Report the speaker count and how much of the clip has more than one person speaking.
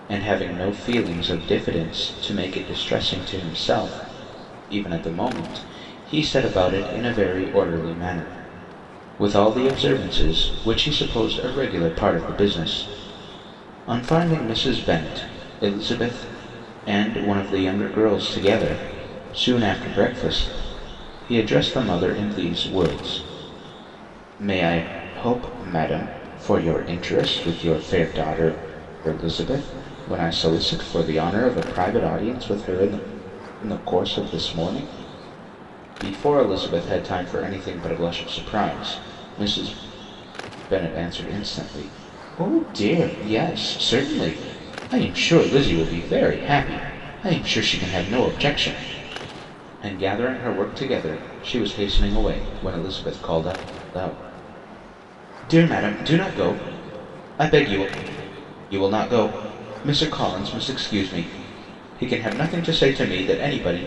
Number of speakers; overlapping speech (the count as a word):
one, no overlap